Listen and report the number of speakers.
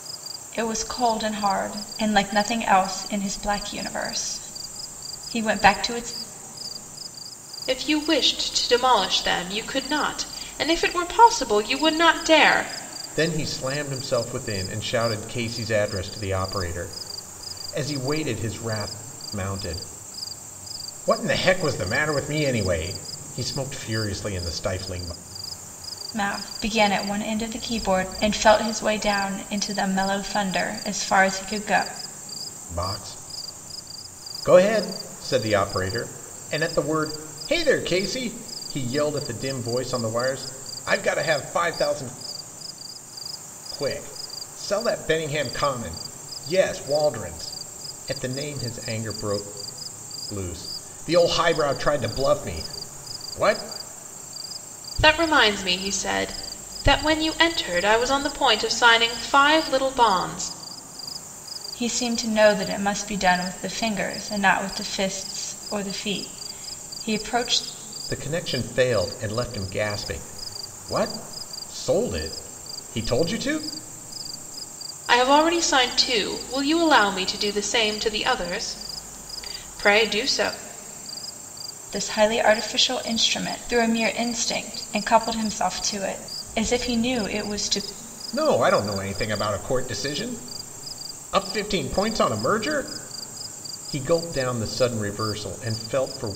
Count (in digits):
3